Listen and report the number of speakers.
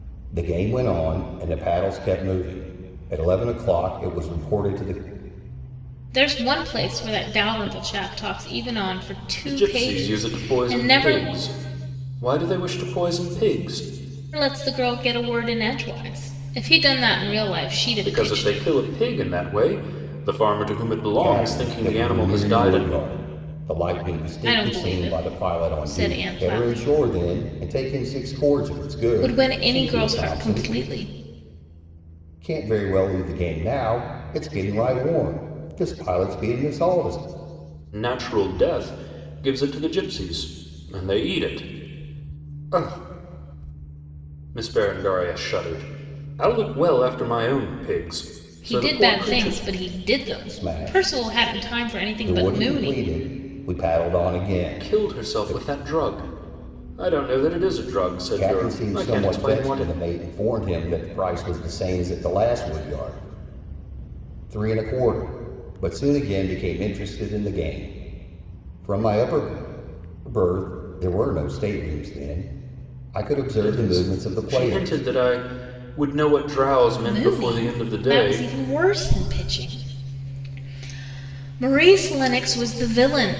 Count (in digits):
3